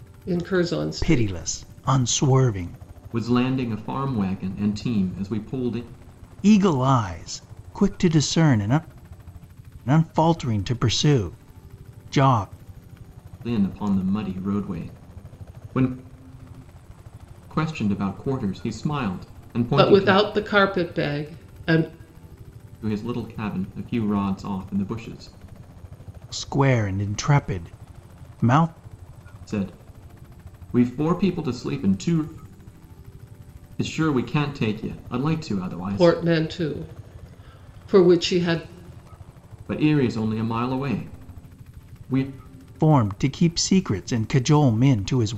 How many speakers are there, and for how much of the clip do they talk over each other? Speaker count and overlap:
three, about 3%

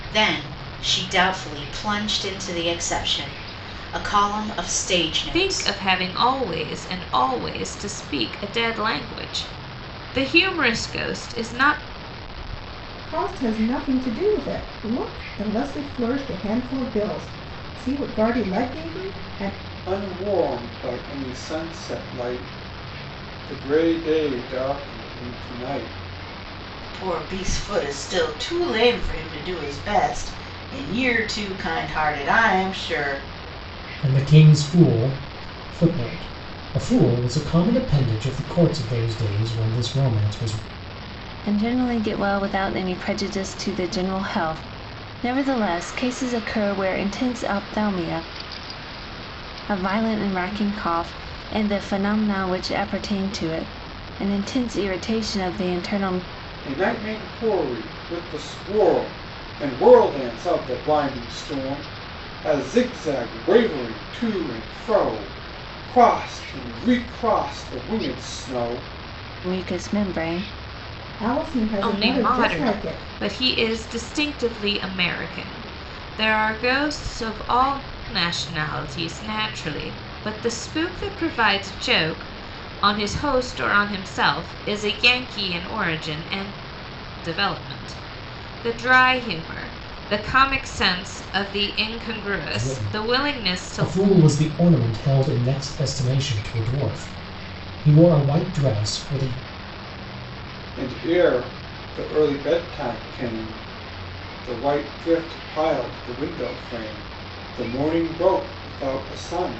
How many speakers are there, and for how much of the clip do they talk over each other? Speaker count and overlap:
seven, about 3%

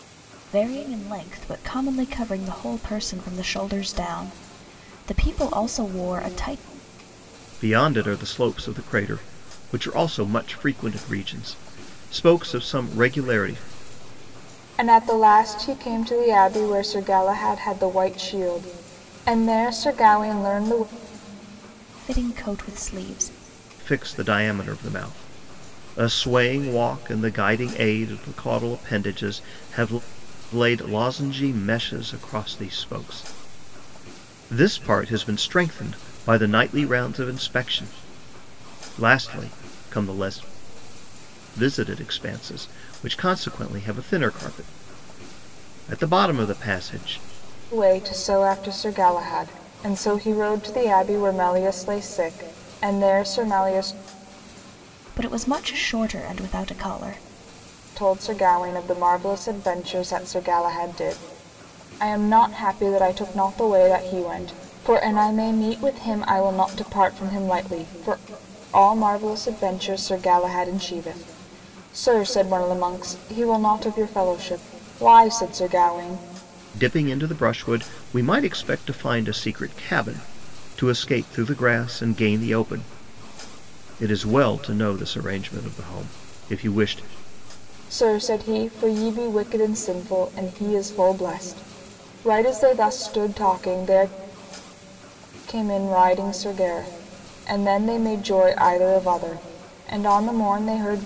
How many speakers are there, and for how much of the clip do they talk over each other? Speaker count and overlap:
three, no overlap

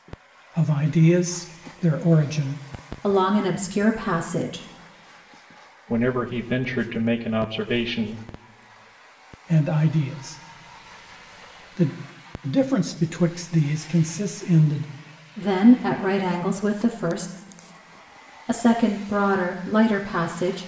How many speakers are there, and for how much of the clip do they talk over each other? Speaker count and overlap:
three, no overlap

